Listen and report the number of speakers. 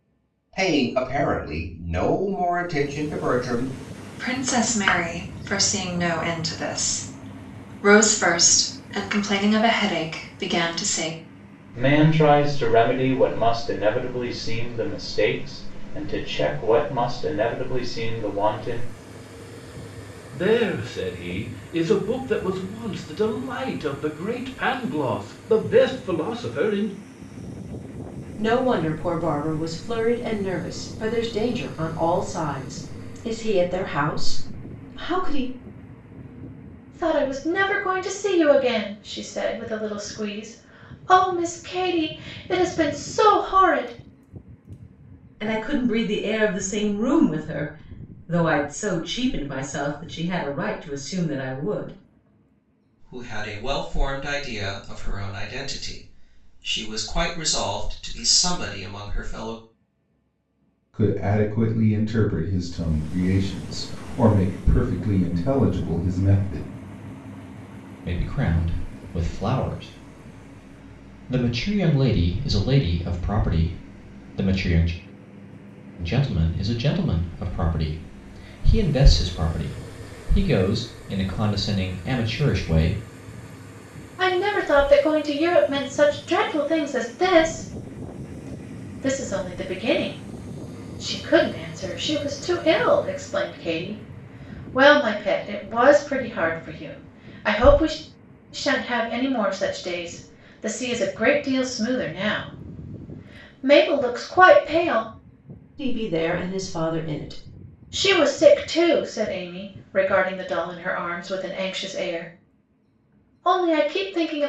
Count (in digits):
10